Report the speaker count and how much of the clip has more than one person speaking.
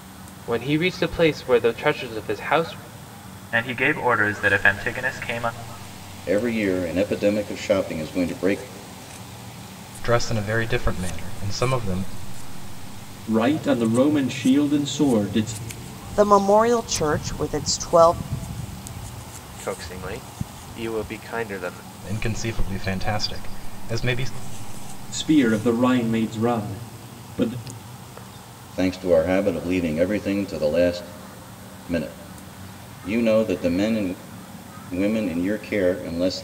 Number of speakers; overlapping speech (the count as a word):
seven, no overlap